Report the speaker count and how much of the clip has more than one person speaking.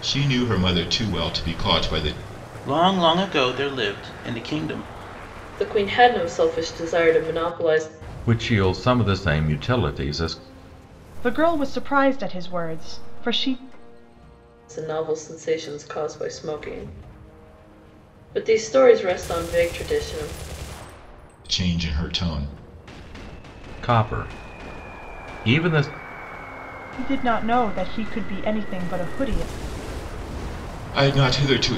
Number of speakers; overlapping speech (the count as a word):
five, no overlap